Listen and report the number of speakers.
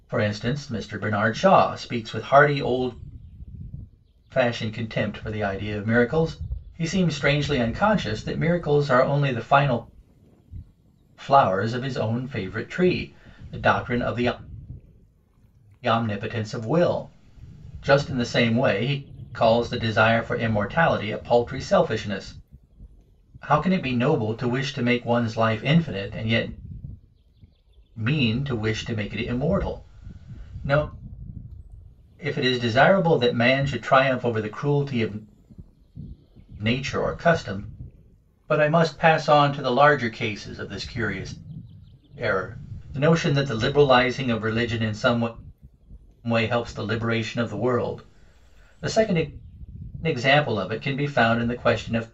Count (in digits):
1